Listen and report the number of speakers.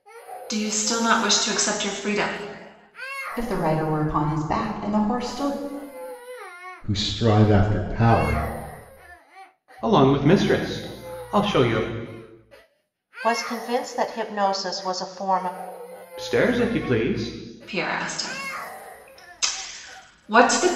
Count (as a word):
five